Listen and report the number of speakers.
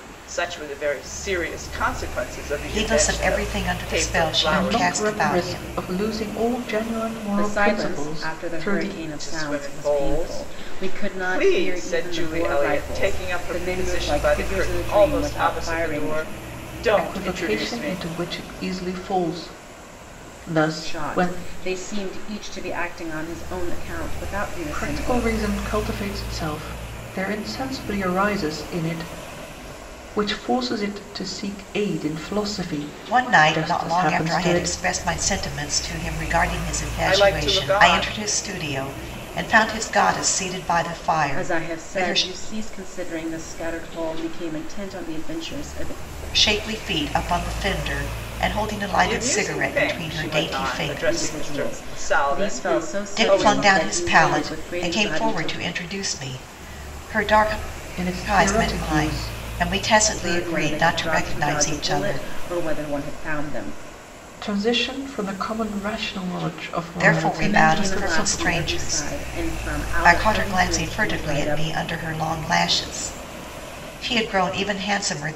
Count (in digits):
4